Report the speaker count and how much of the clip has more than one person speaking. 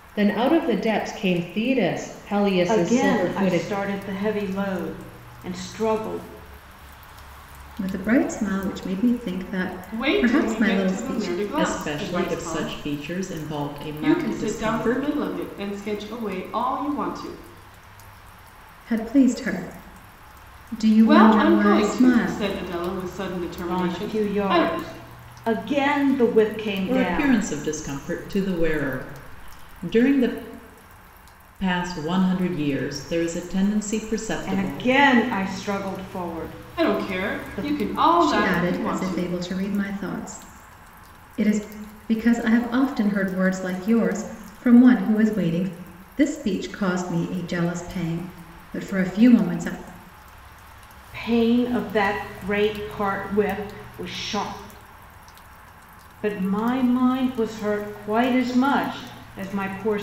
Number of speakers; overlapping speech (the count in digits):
5, about 17%